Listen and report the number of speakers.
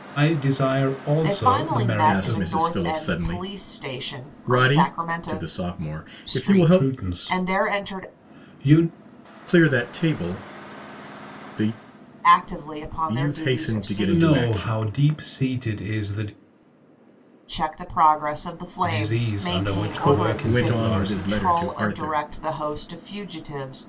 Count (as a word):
three